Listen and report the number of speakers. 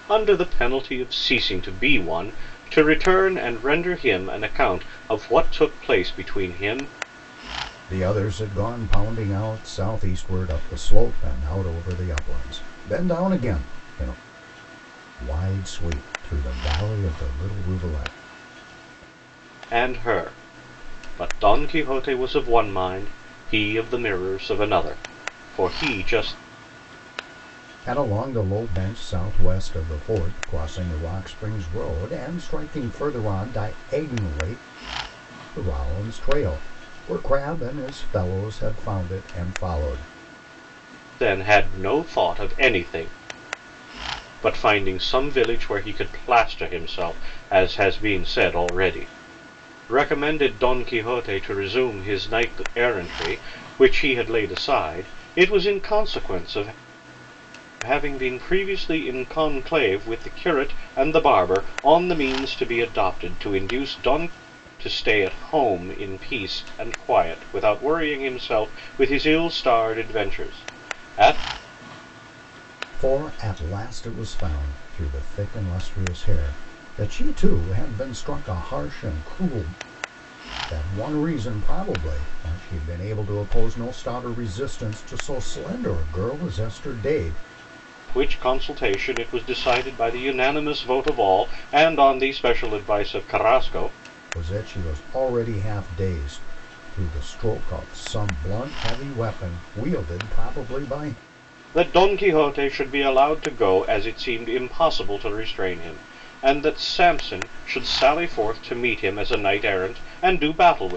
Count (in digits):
2